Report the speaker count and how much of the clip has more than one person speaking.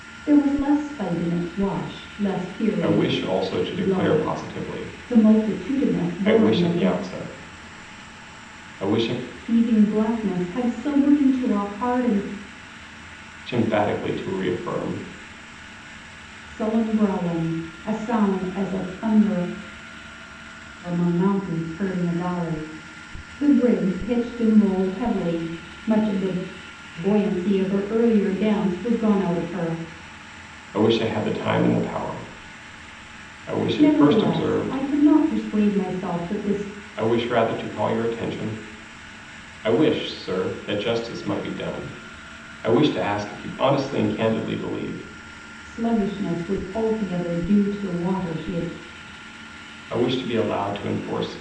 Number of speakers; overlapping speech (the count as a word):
two, about 7%